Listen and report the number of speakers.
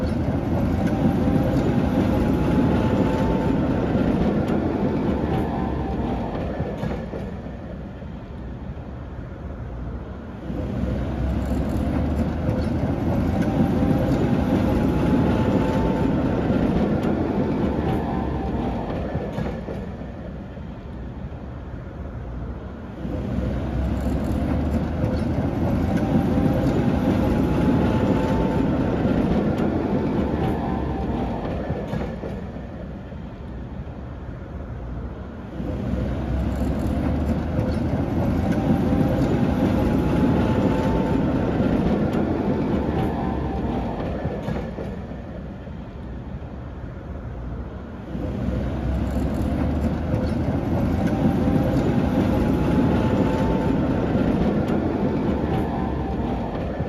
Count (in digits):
0